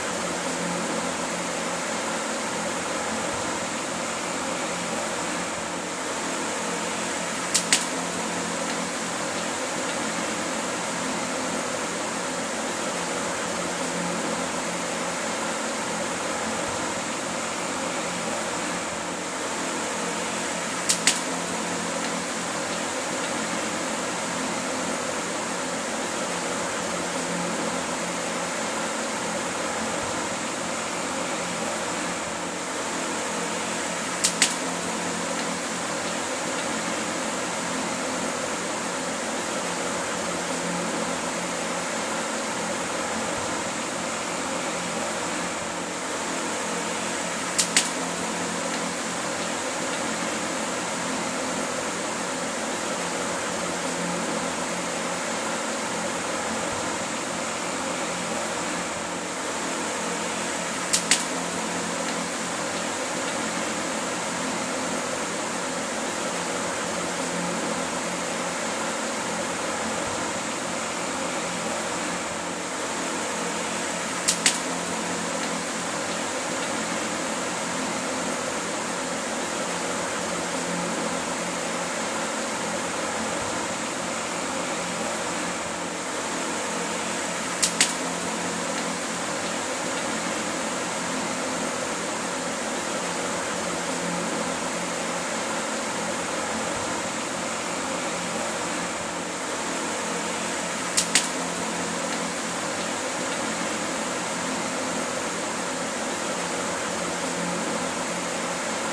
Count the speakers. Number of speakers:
zero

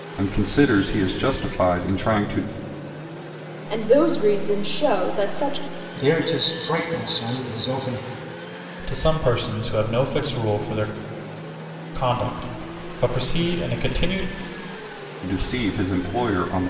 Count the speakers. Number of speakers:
four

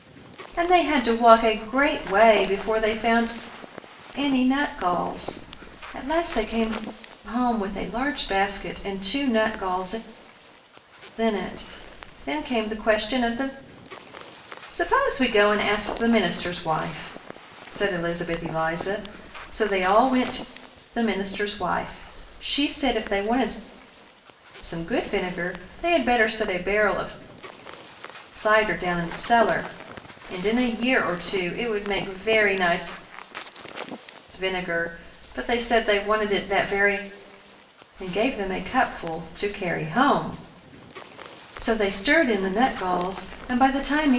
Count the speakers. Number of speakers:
one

